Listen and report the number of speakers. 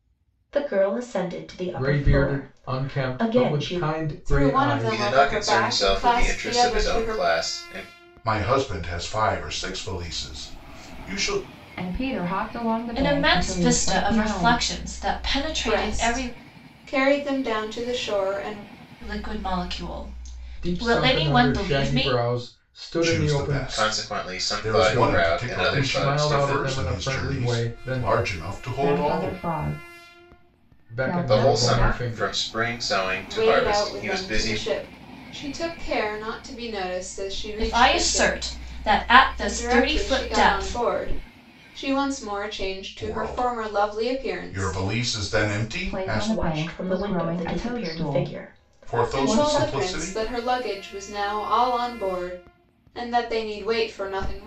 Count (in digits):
7